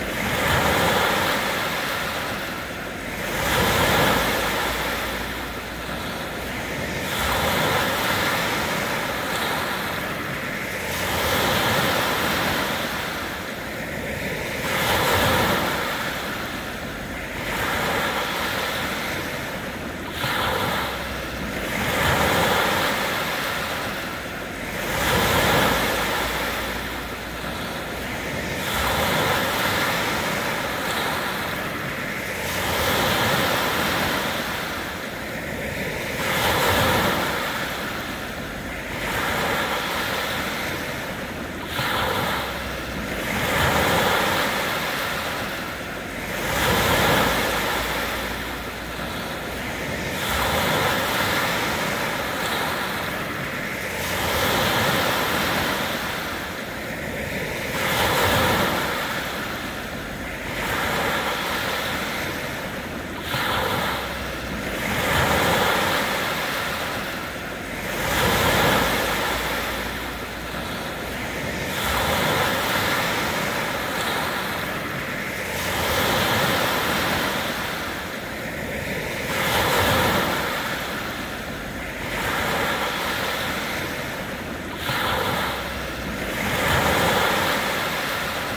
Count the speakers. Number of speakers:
zero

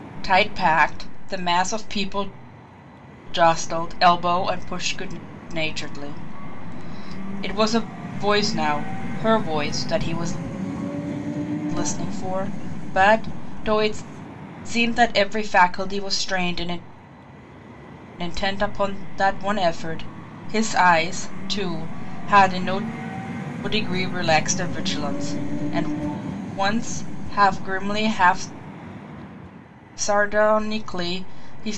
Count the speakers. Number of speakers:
one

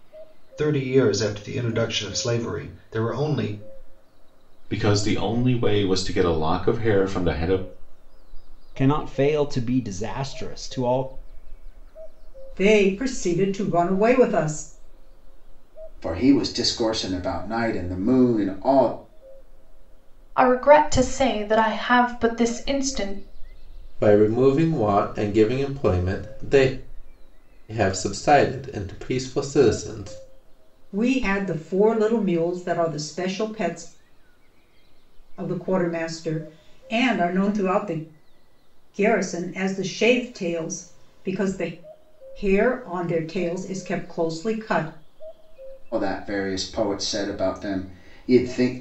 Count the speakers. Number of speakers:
seven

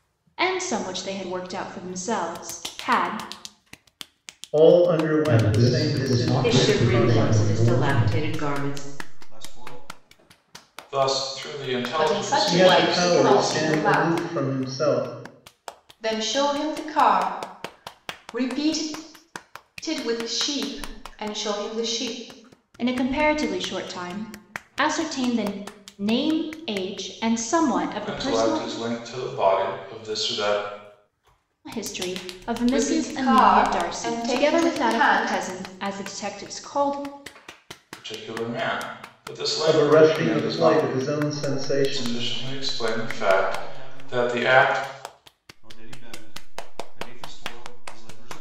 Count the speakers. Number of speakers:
seven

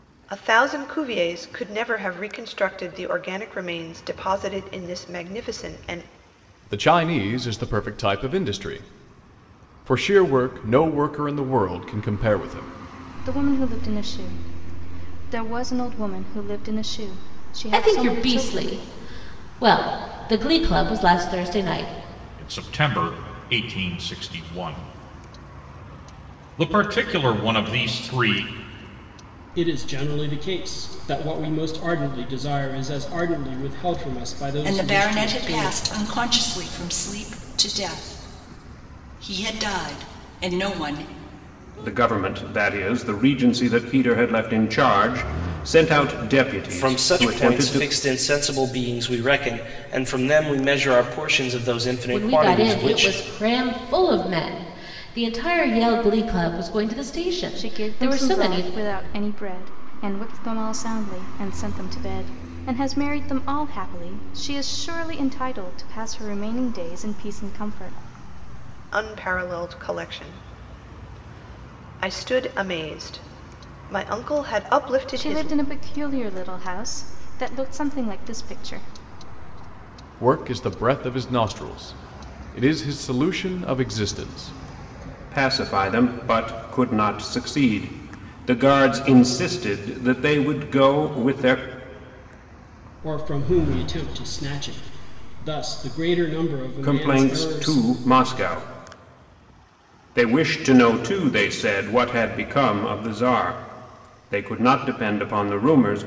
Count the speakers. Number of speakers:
nine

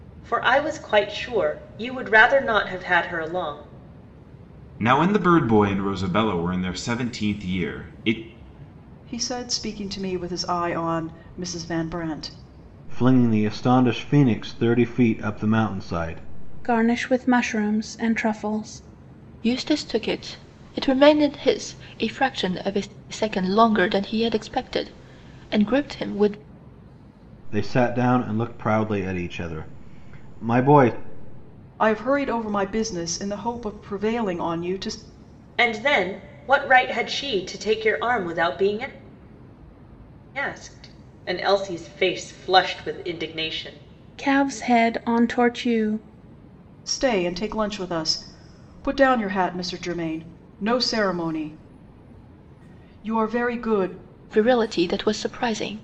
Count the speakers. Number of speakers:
six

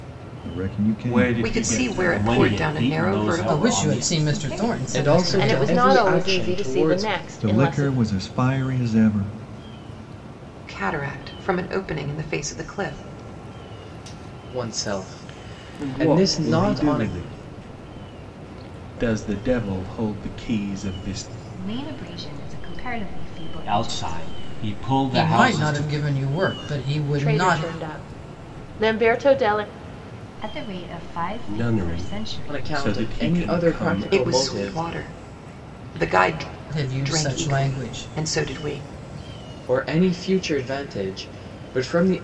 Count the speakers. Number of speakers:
eight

